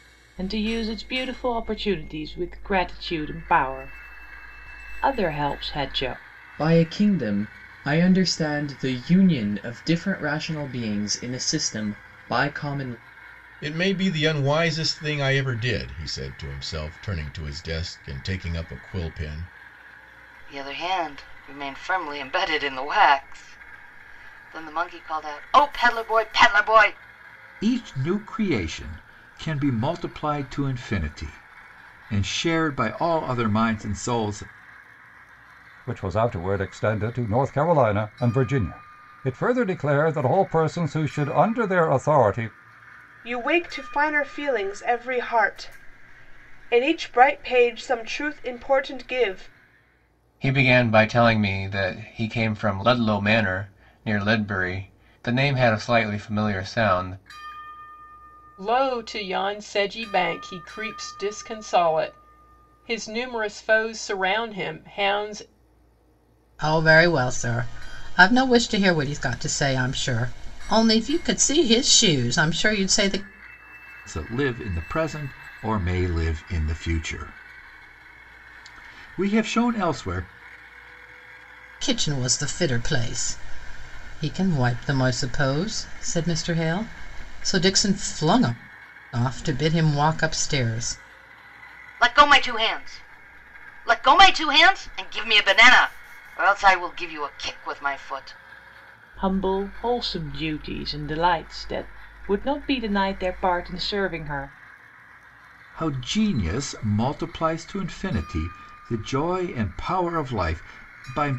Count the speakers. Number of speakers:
ten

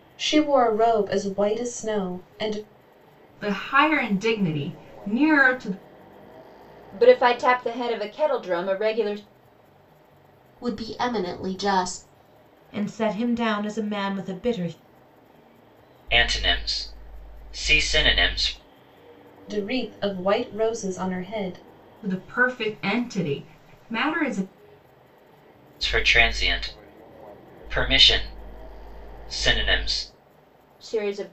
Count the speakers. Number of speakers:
six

